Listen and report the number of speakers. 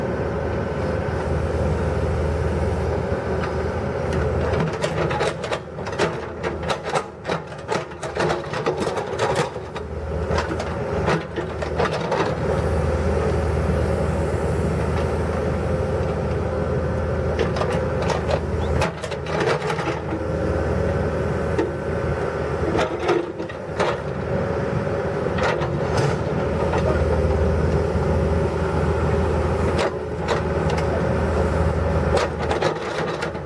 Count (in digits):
0